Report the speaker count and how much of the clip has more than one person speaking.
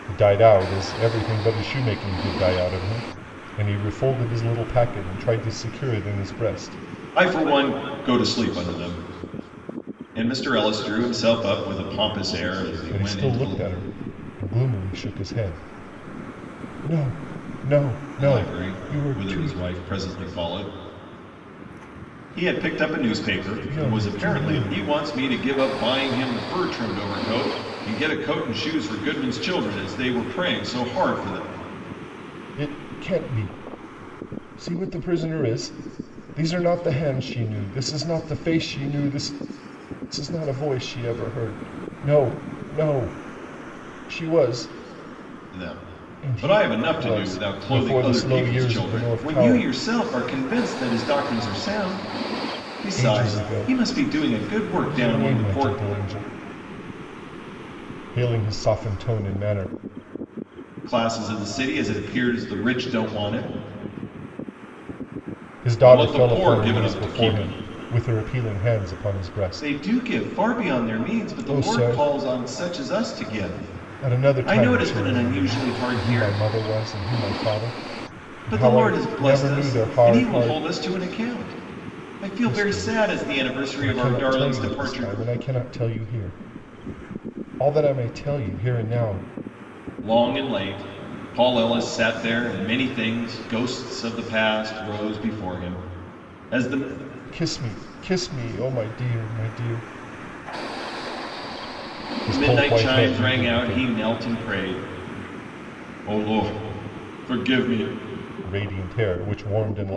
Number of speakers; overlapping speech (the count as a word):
two, about 21%